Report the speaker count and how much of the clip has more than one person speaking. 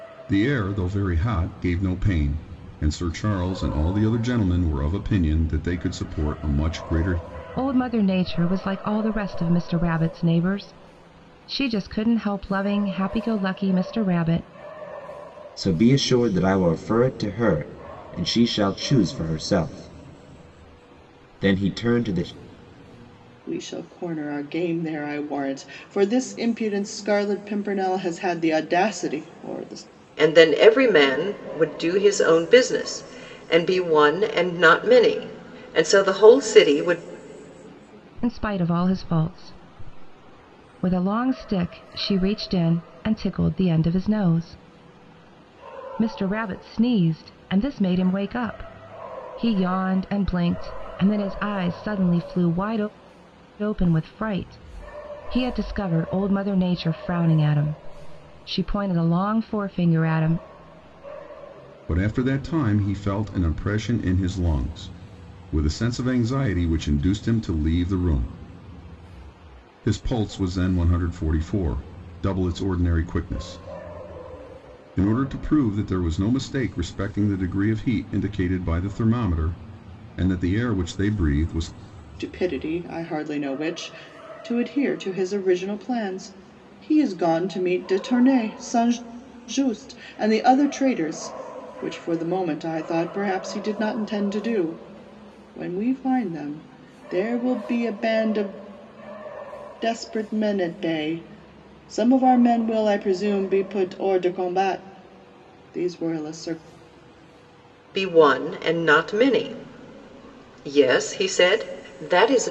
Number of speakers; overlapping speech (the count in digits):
5, no overlap